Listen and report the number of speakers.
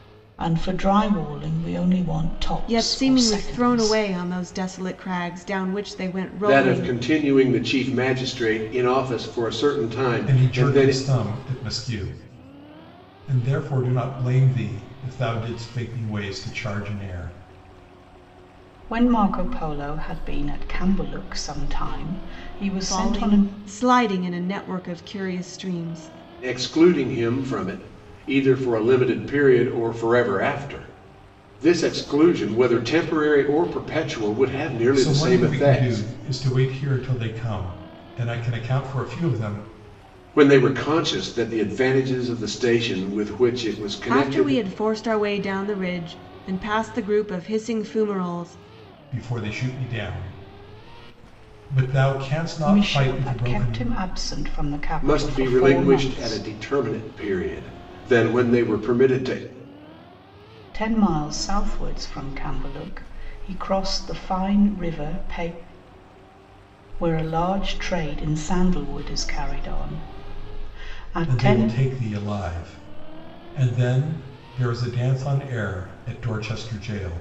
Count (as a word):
four